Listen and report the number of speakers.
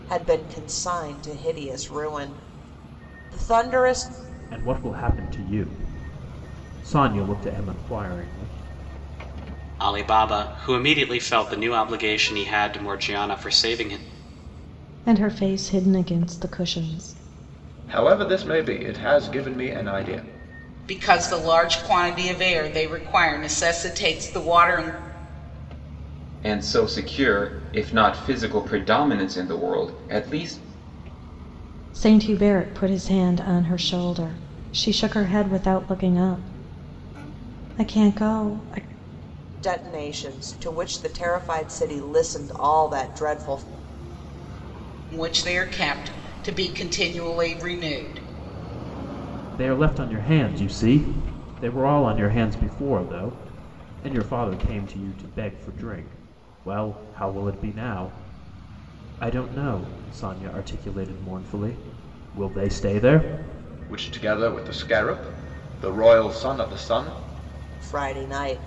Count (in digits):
7